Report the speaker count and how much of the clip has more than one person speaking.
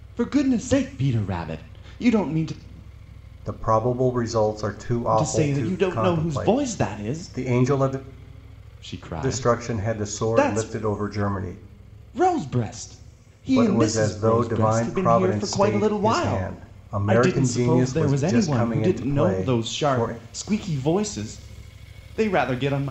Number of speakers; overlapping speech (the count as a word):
two, about 43%